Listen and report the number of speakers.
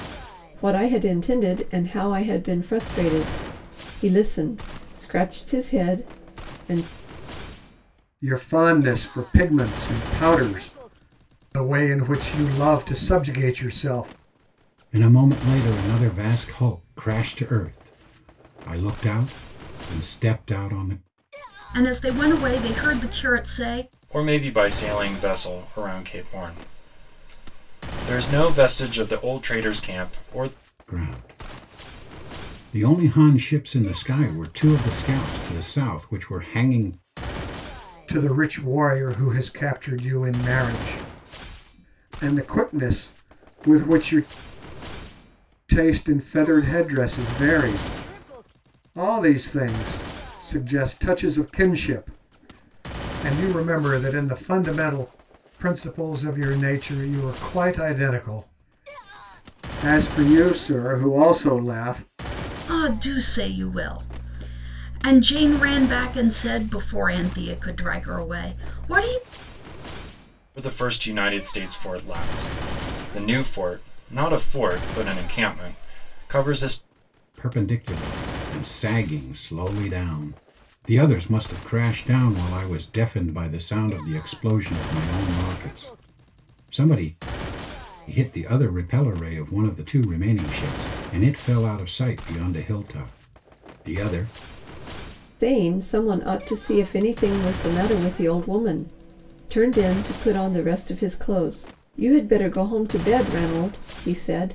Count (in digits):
5